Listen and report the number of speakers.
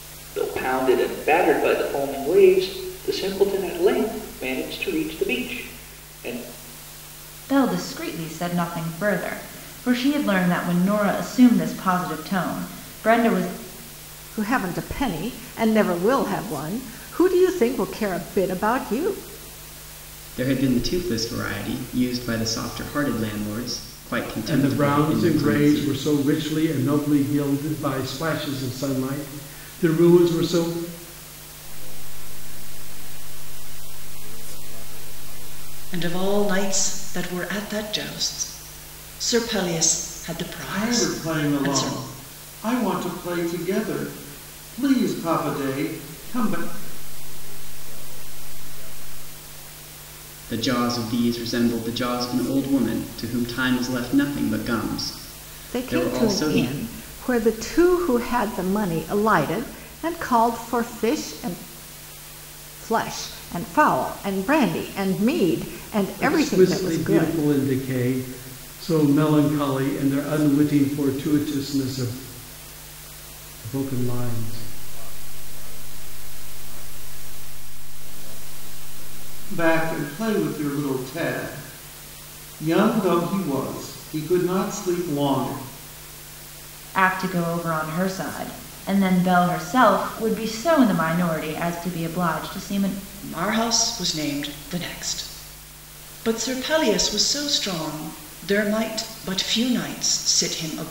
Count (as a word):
eight